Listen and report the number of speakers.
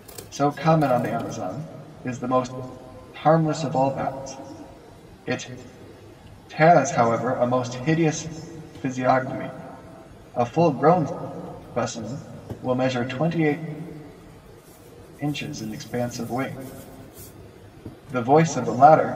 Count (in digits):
1